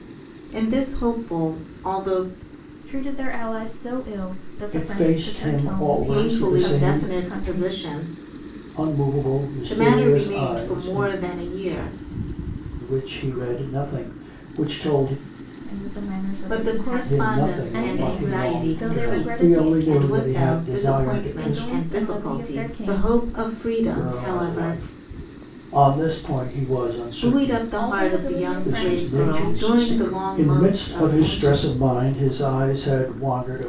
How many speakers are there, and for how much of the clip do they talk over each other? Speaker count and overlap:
3, about 49%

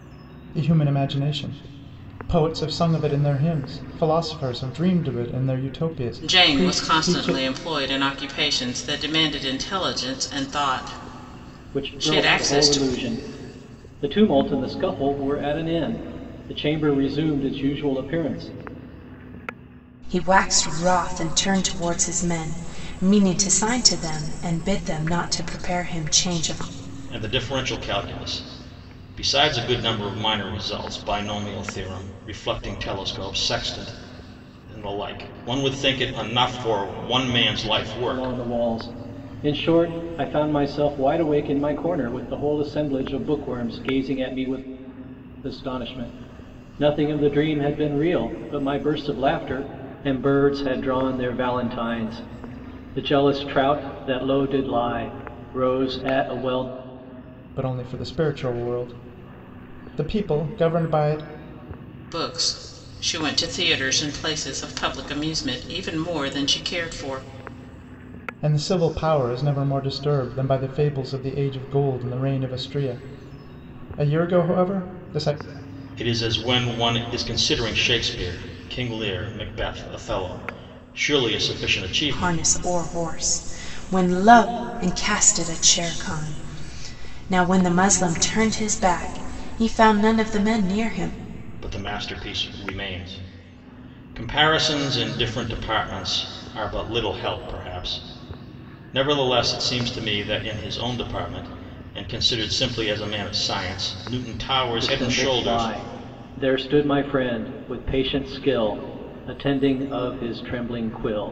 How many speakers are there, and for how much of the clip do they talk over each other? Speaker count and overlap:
5, about 4%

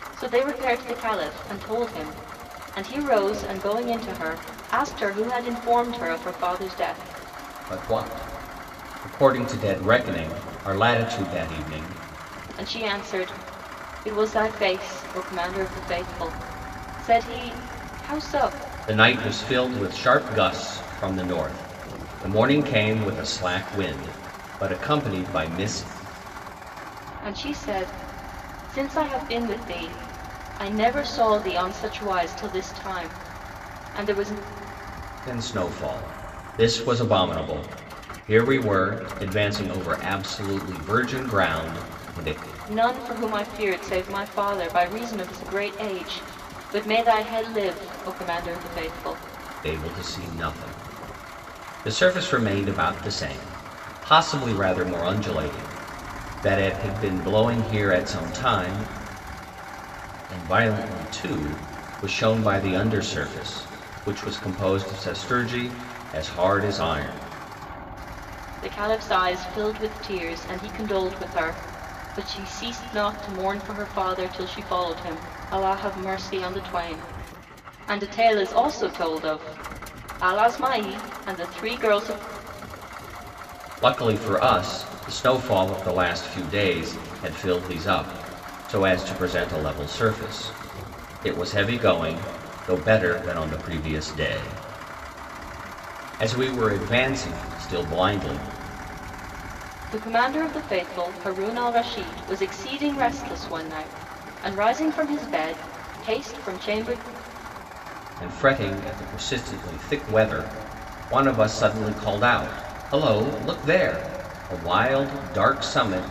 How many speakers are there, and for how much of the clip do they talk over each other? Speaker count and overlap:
2, no overlap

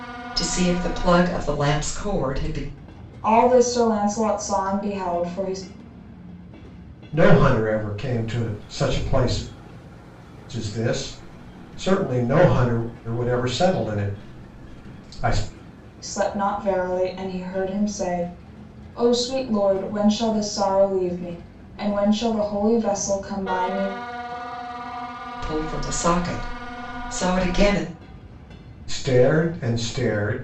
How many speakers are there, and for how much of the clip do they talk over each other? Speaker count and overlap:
3, no overlap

